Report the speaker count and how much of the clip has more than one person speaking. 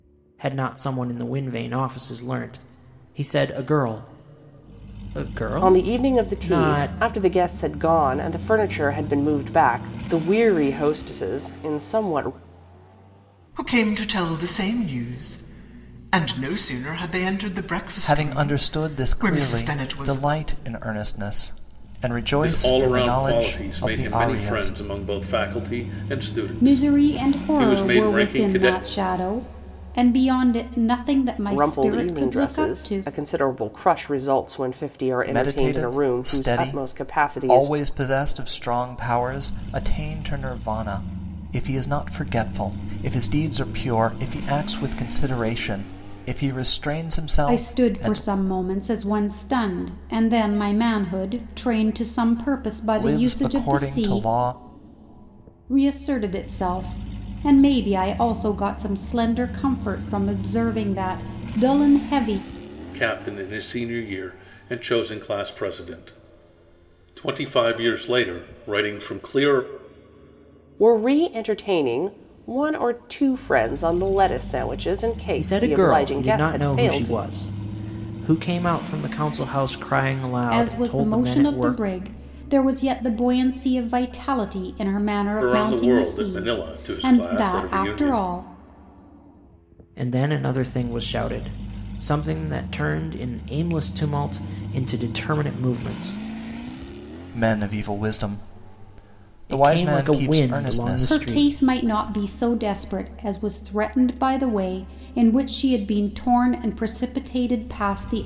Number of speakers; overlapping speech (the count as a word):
six, about 21%